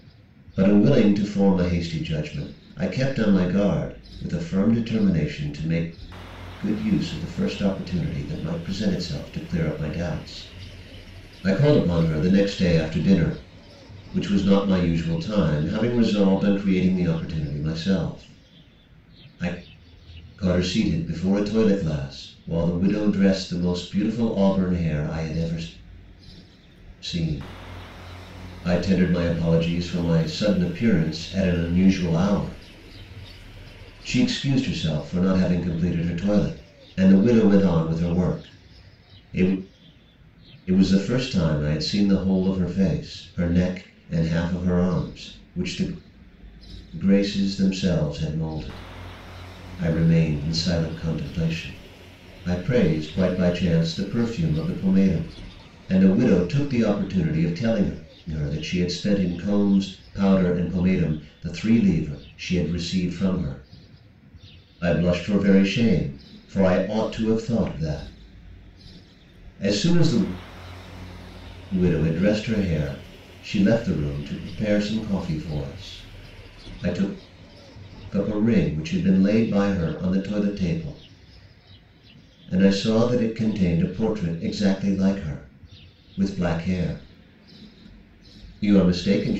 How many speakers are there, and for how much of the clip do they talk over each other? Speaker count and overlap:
one, no overlap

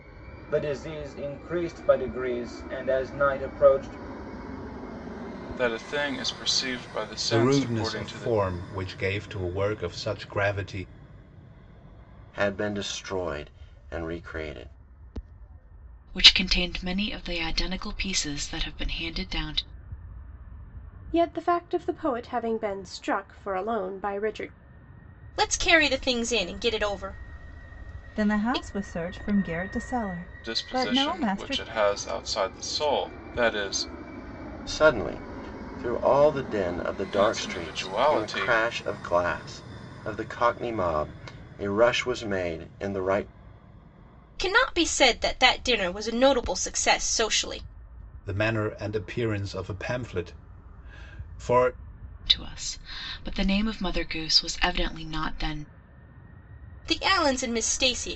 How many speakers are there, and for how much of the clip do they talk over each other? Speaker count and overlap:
eight, about 8%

